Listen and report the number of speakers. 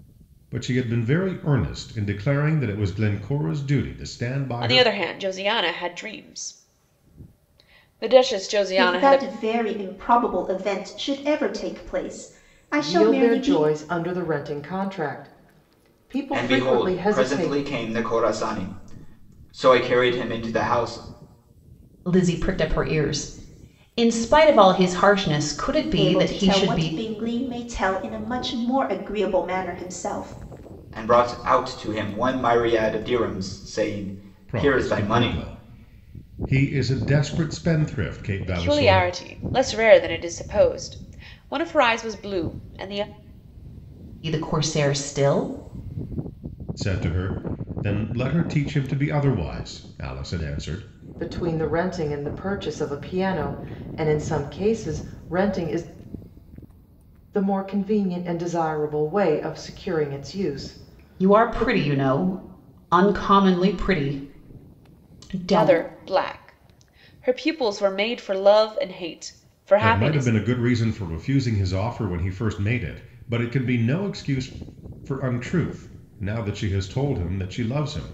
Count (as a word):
six